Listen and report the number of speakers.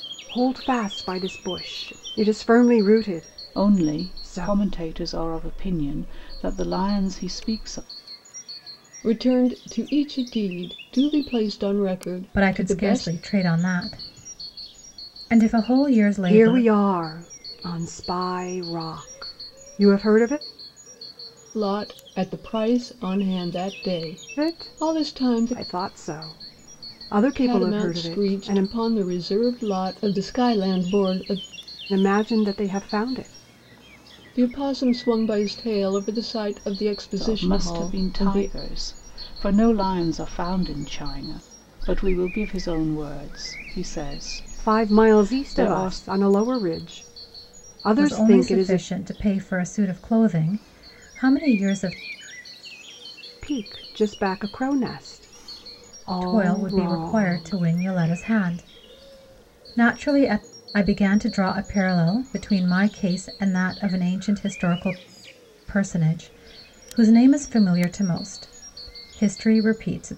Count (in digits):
4